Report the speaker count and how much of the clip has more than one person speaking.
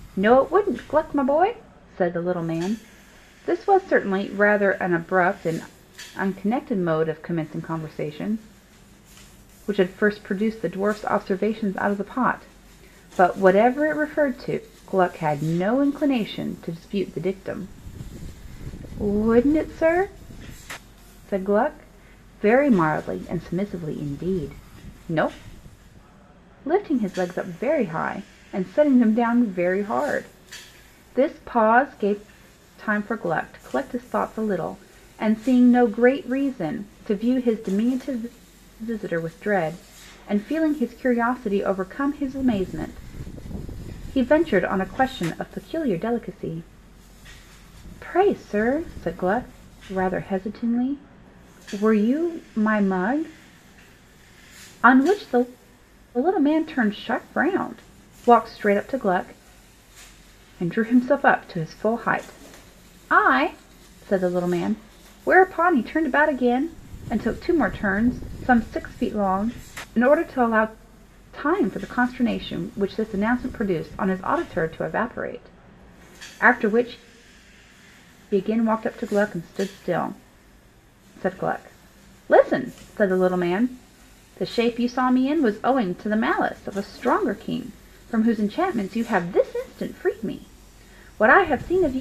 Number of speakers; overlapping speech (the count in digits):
1, no overlap